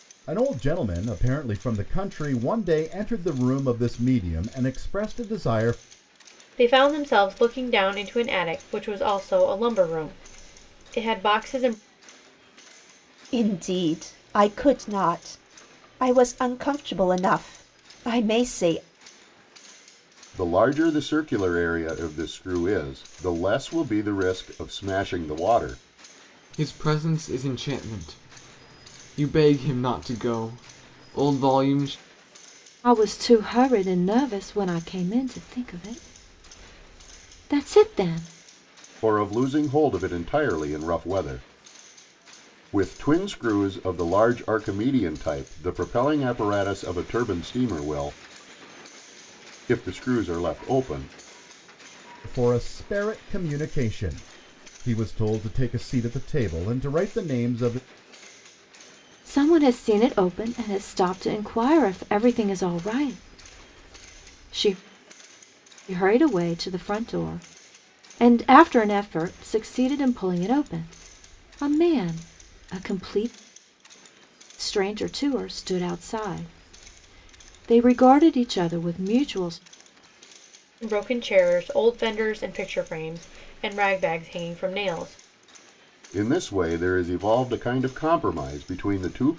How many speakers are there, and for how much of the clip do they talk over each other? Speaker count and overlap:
6, no overlap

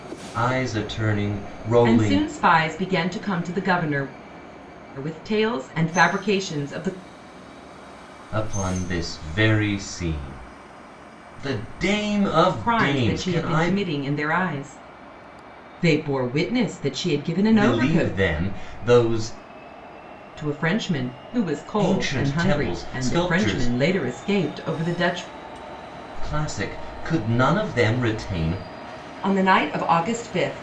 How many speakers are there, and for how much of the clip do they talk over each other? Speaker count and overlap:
2, about 14%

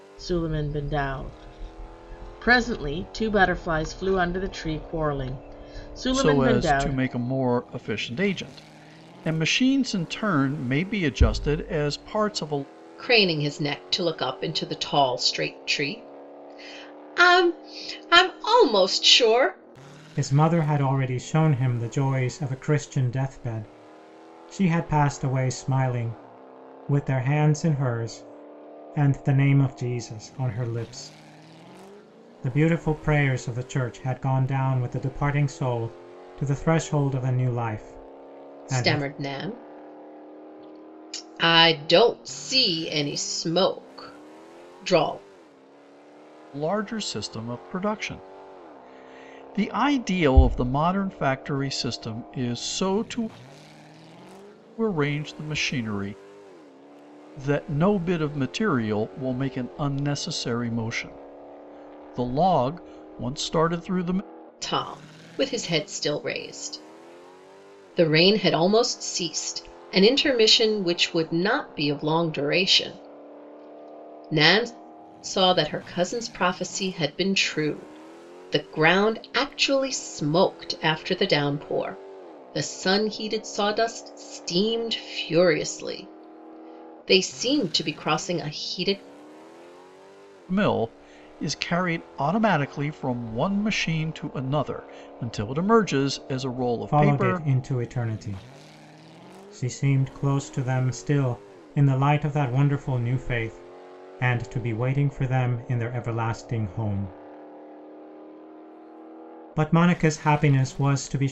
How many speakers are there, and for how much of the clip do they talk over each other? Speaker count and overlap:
4, about 2%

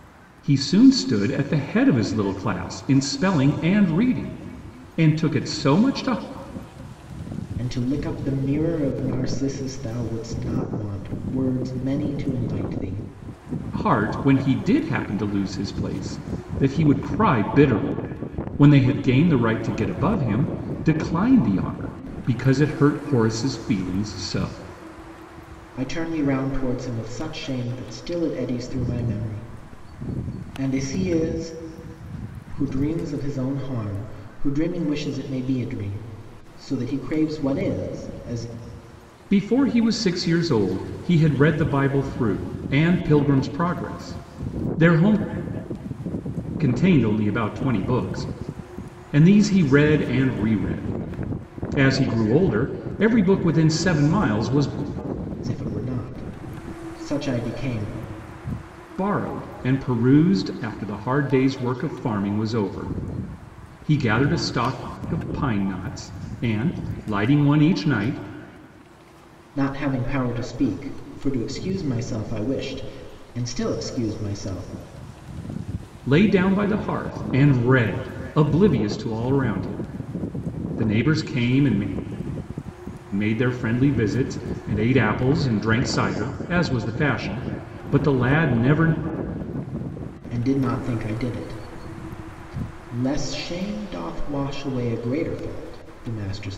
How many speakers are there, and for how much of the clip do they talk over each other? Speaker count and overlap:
2, no overlap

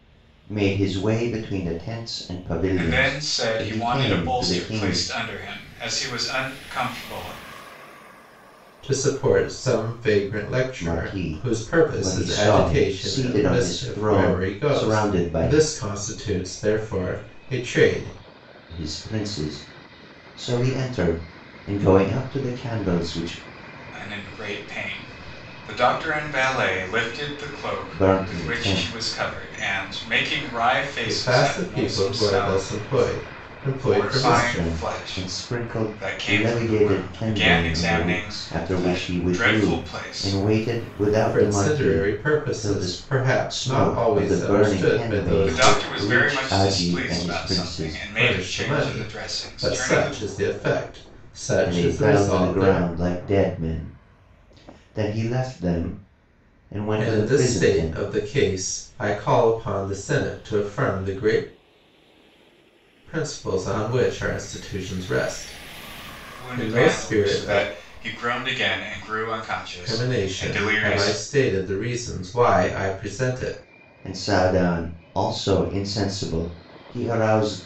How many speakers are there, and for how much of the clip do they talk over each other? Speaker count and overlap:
3, about 38%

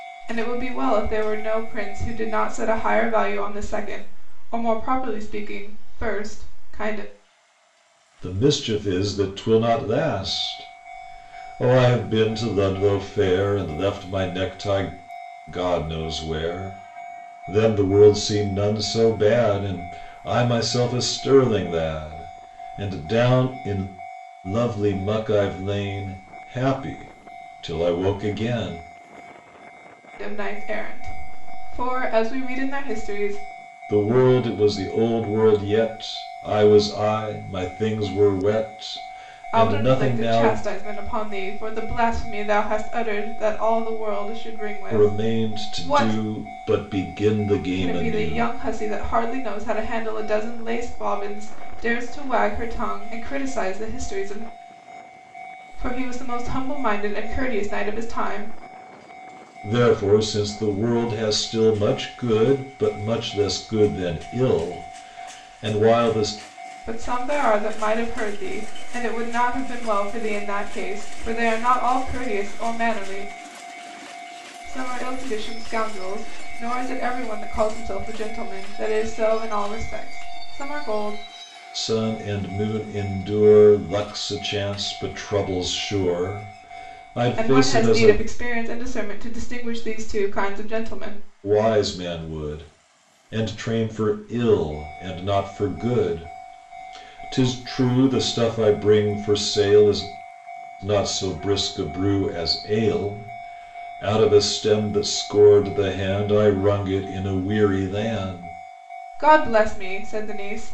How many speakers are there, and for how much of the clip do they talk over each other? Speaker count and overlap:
2, about 4%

